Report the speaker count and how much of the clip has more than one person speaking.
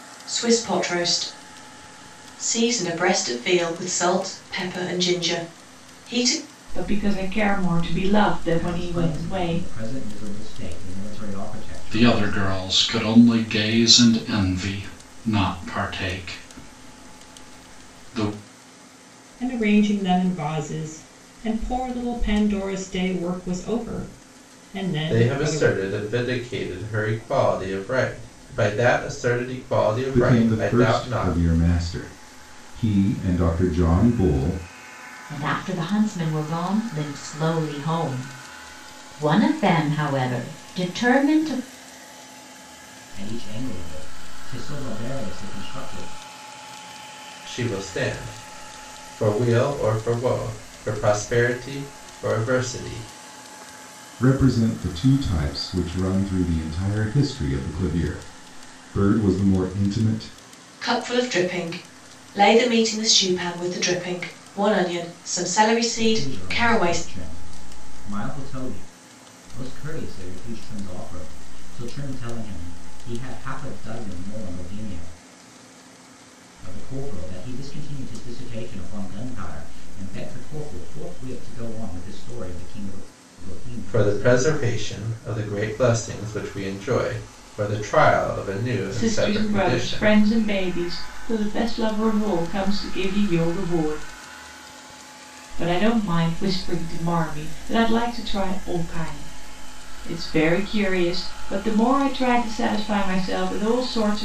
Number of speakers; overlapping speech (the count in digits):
8, about 7%